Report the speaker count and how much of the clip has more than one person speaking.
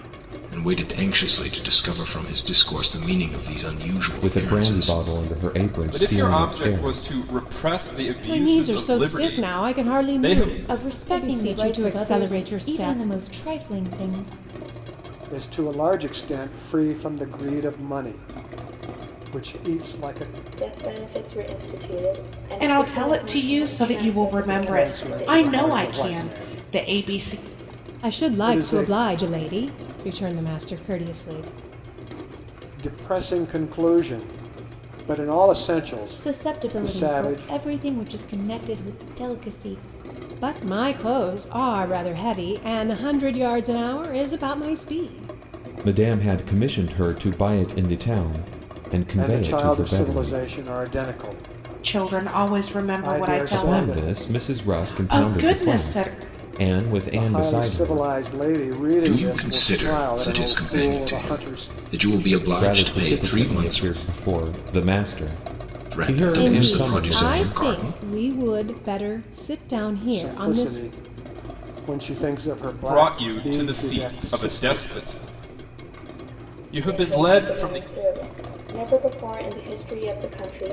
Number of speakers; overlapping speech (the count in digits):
8, about 38%